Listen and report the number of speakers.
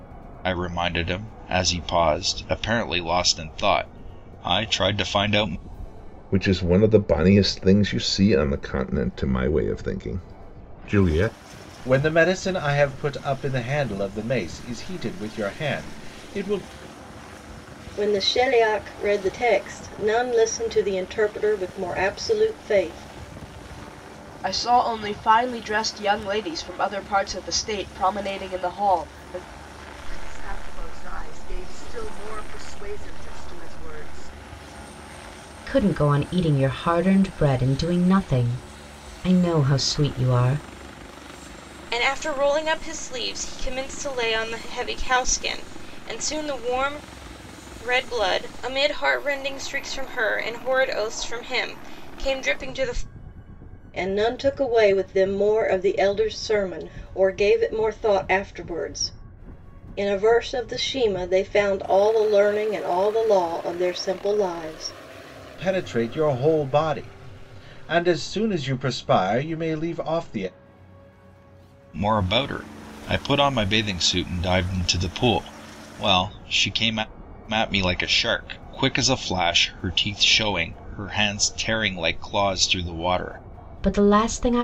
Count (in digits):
8